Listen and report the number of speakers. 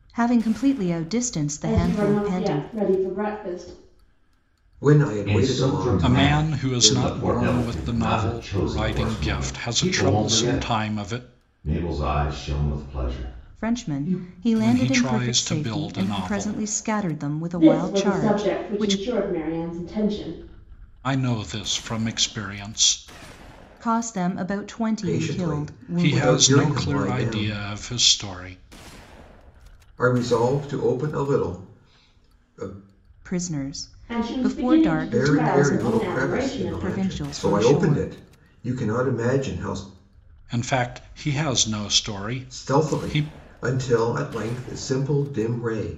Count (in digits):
5